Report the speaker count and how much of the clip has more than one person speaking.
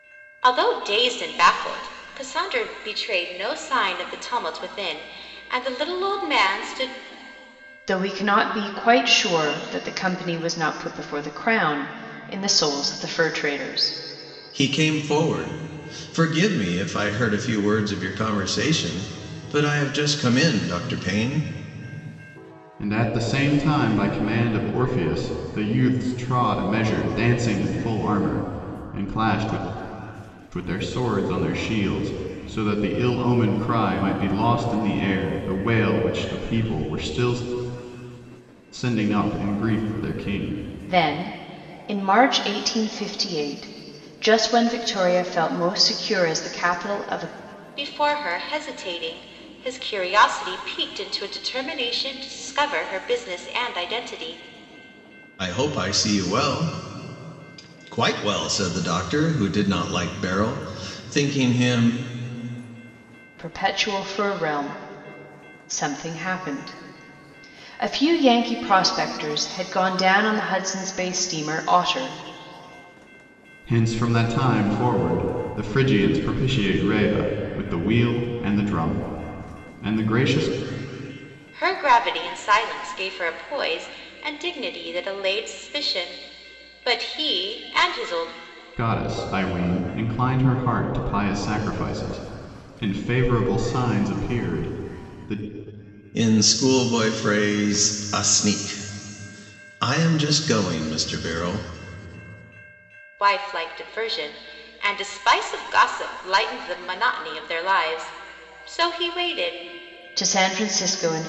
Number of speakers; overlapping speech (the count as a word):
four, no overlap